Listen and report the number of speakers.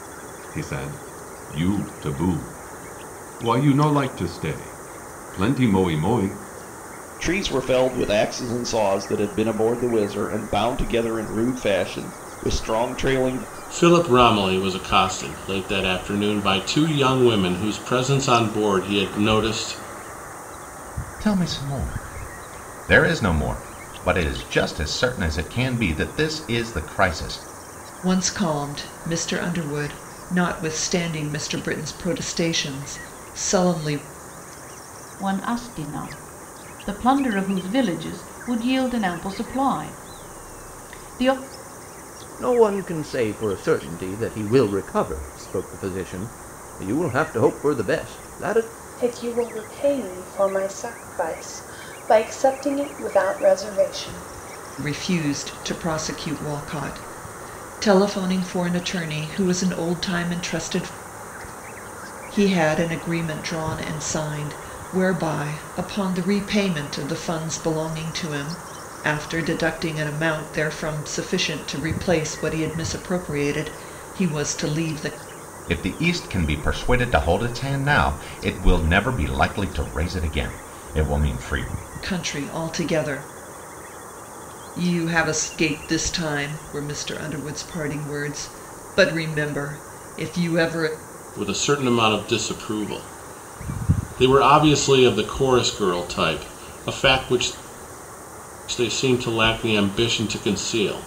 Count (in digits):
8